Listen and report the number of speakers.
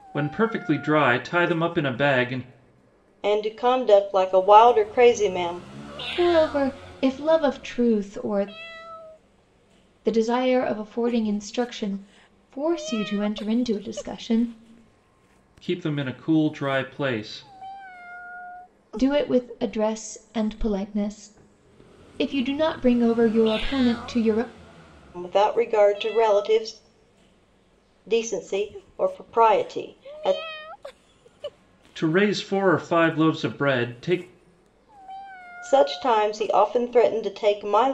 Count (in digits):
3